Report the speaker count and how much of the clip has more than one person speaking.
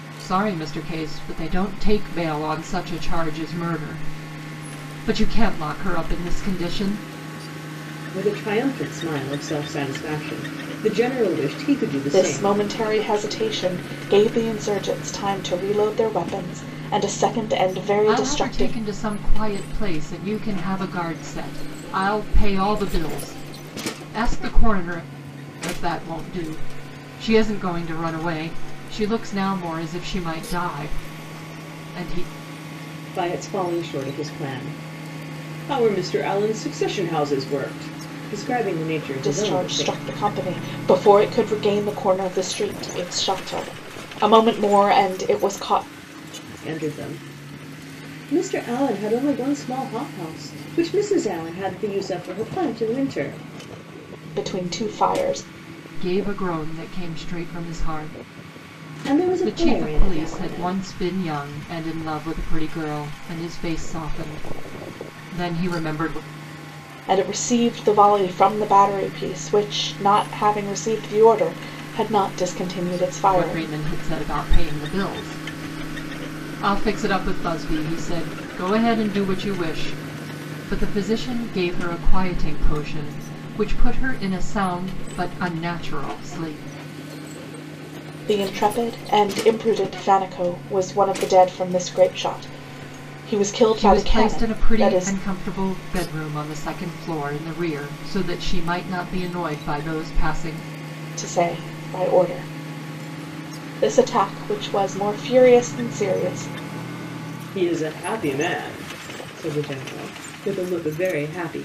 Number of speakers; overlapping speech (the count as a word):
three, about 5%